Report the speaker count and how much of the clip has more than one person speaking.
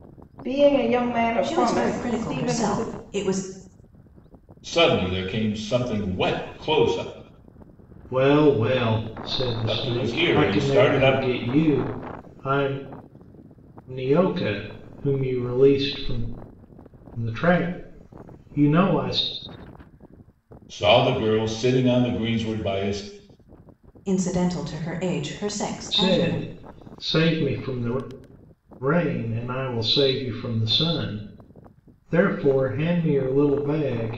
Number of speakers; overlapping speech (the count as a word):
four, about 10%